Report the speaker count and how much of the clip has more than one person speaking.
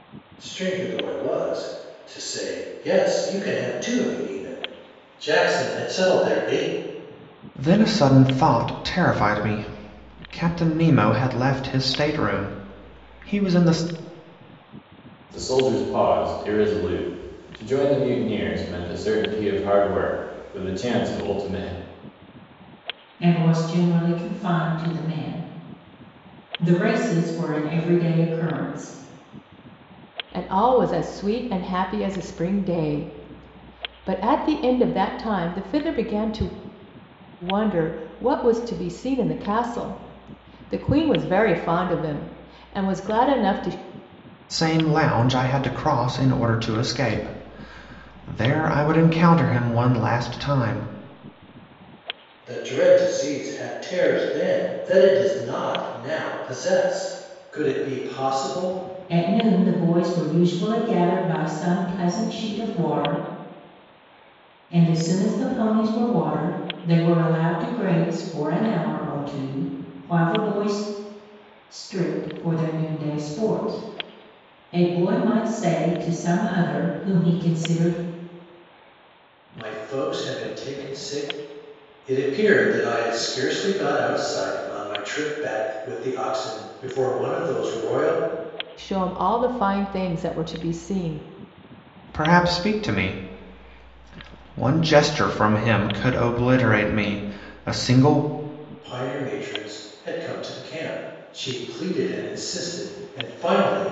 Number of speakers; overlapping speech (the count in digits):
5, no overlap